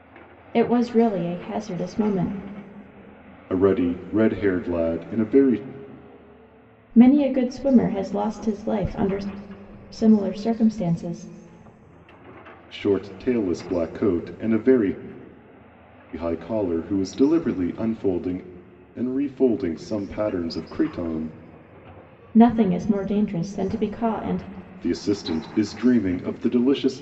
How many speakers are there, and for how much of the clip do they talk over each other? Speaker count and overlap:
2, no overlap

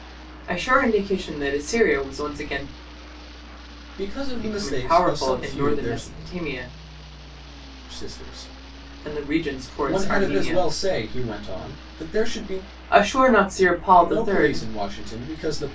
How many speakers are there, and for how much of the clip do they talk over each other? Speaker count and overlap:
2, about 25%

